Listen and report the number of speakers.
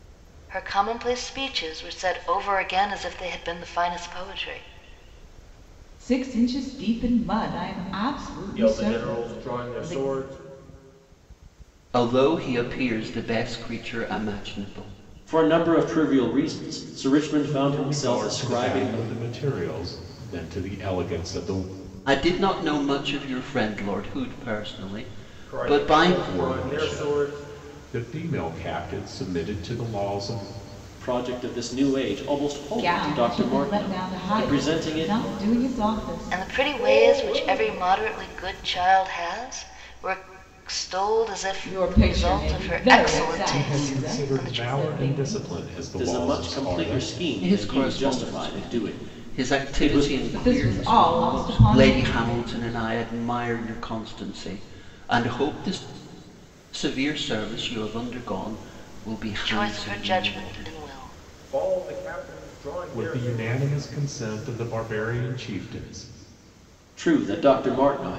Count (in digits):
6